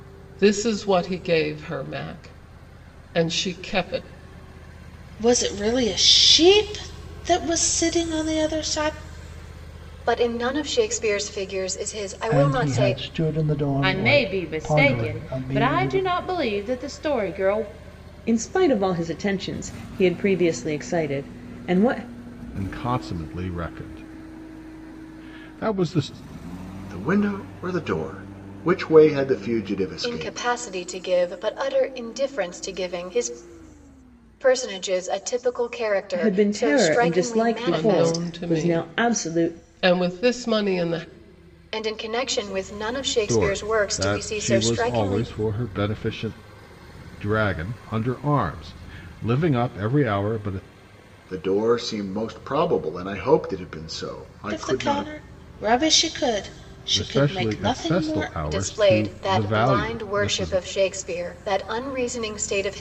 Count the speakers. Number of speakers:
8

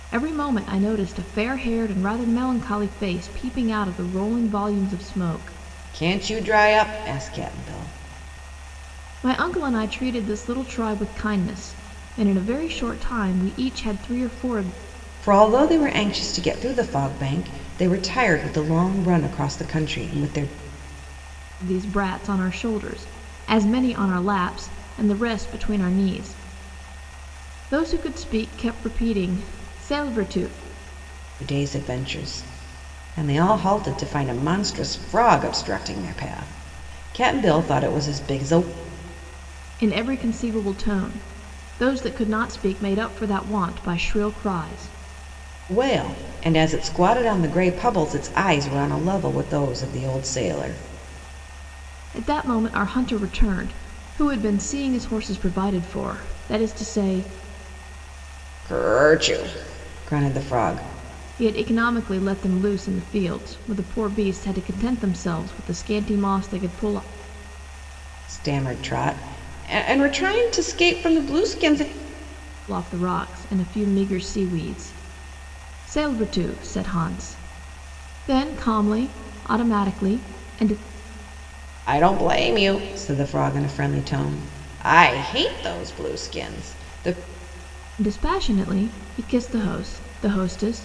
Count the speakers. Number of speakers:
2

